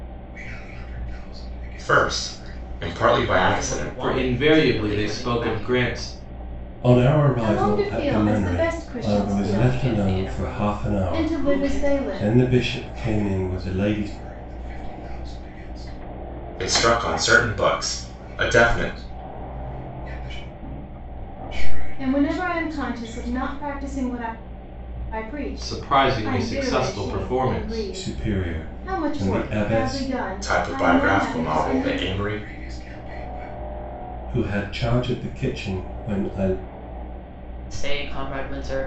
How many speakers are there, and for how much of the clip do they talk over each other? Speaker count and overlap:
6, about 49%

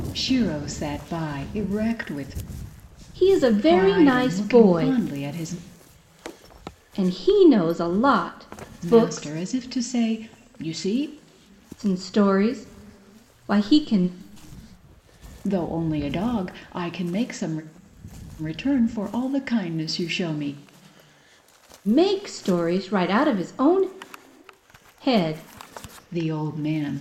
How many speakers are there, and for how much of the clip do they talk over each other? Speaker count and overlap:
2, about 7%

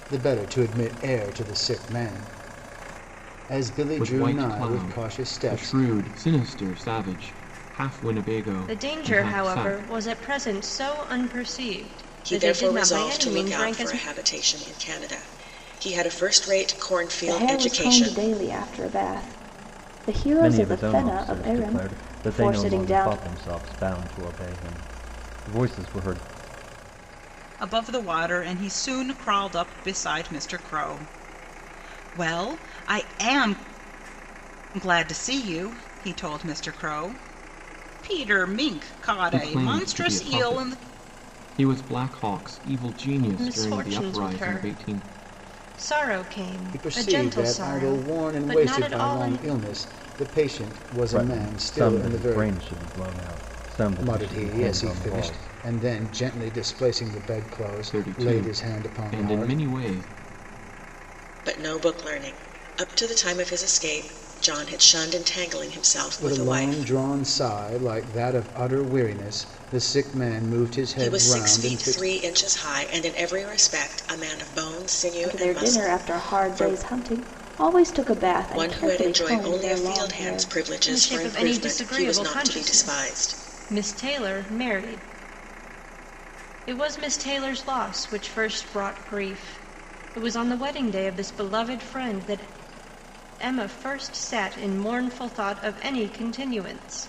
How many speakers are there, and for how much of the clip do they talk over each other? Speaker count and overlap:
7, about 29%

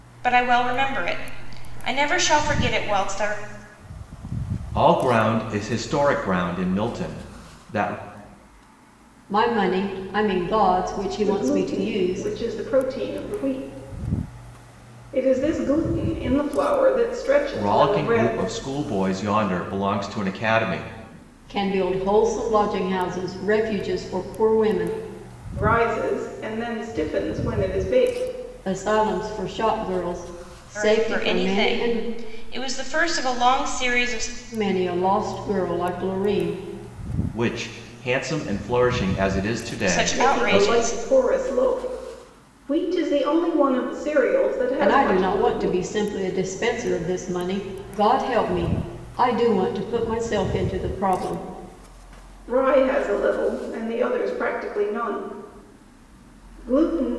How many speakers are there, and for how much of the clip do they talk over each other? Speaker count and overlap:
4, about 9%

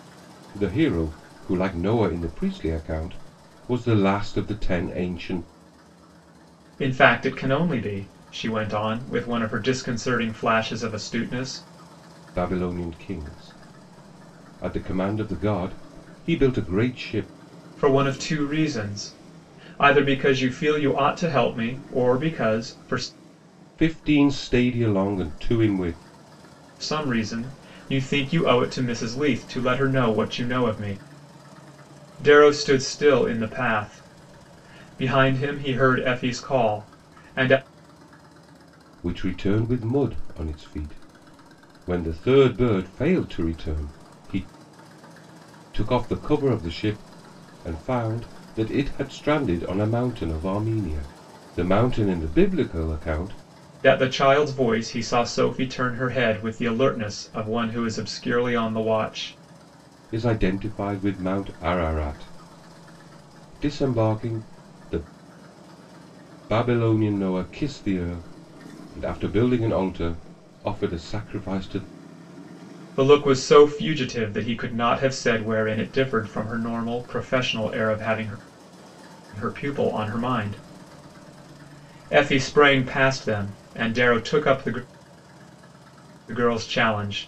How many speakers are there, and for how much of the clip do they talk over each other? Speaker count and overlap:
2, no overlap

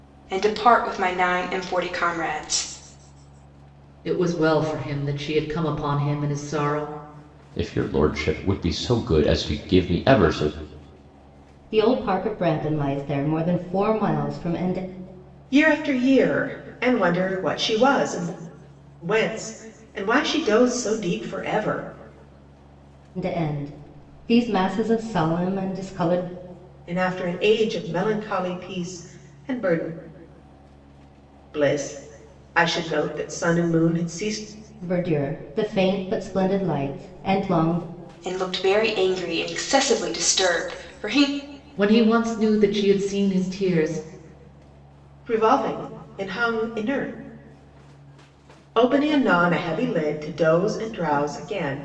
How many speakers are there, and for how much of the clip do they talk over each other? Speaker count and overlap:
5, no overlap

